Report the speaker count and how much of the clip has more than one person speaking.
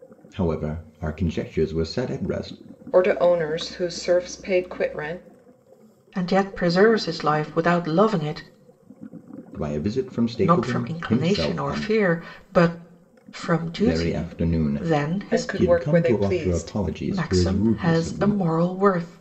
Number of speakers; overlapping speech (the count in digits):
3, about 30%